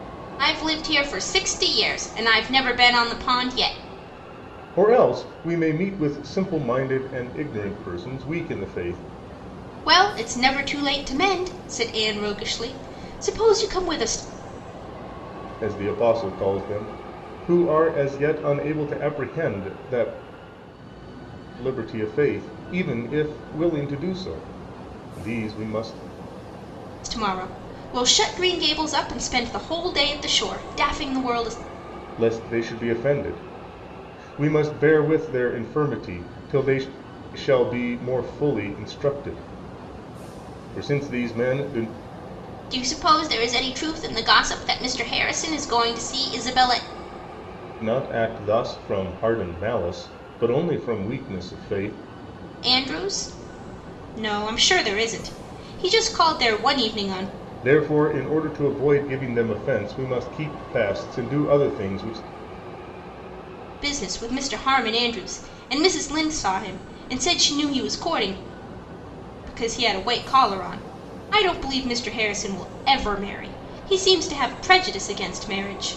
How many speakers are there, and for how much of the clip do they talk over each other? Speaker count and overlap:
two, no overlap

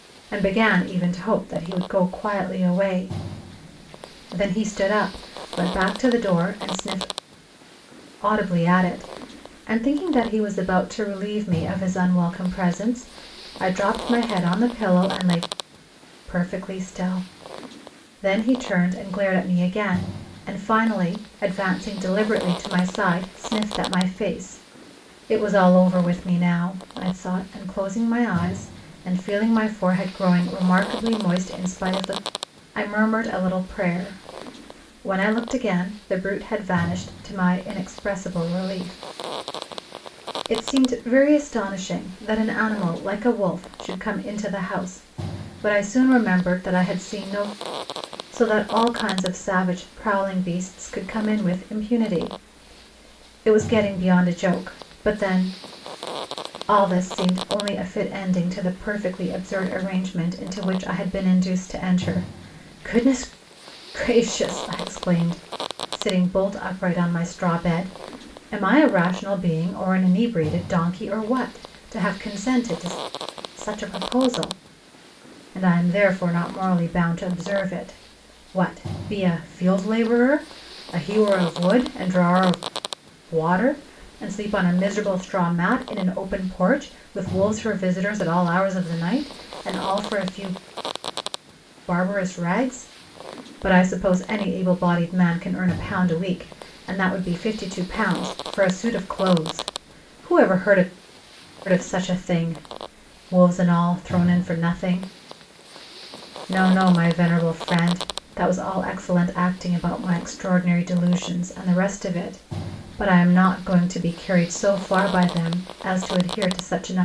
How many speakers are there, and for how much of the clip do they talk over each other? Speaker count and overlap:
one, no overlap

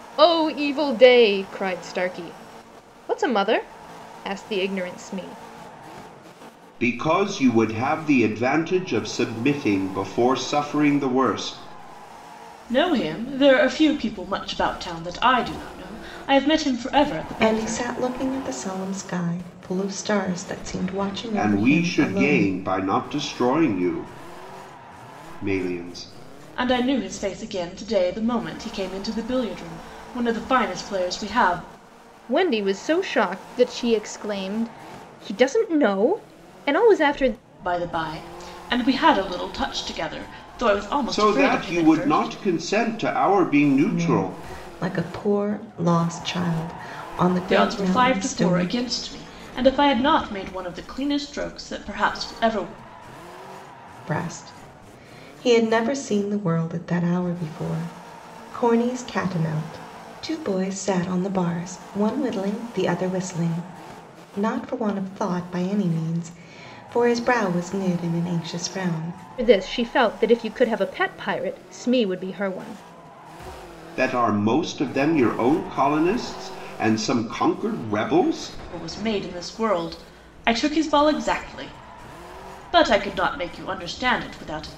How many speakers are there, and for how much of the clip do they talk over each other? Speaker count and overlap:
four, about 6%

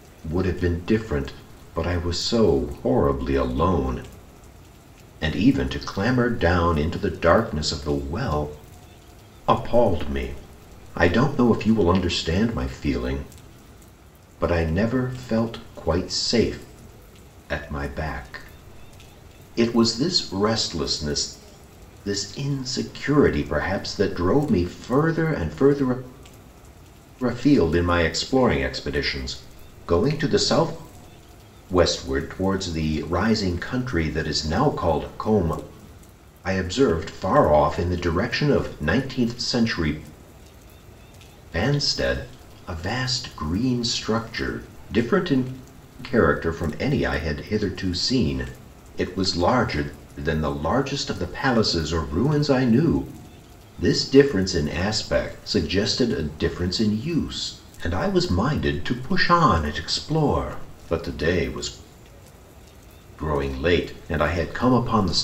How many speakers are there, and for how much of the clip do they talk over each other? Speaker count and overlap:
one, no overlap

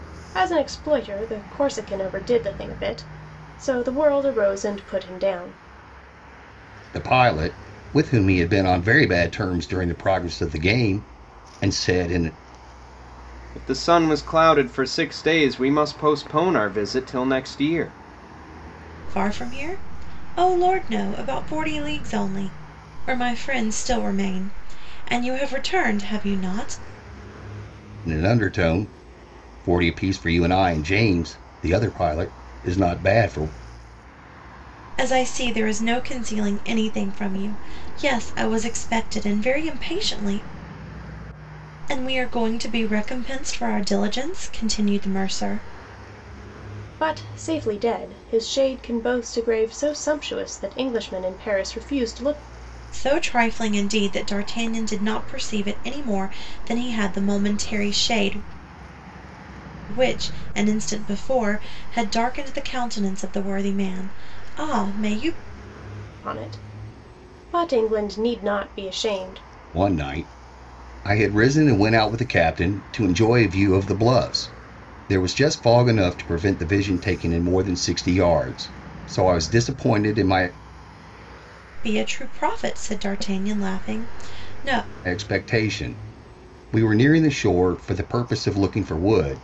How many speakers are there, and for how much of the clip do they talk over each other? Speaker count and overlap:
four, no overlap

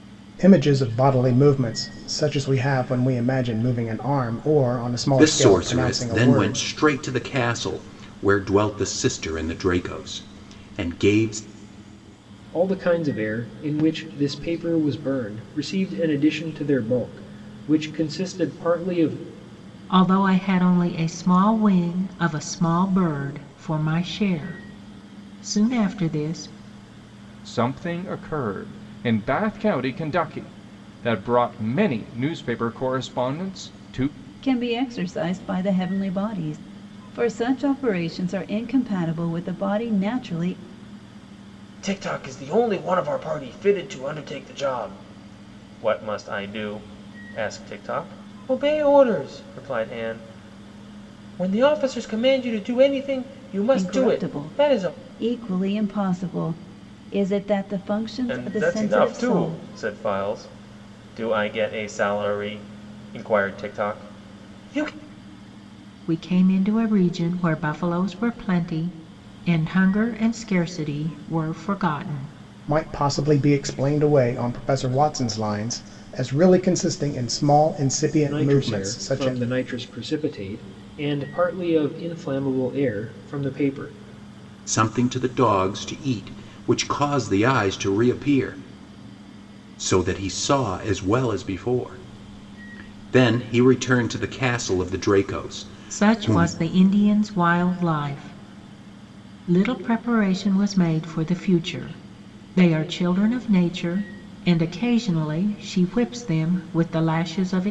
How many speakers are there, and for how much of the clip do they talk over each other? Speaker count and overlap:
seven, about 5%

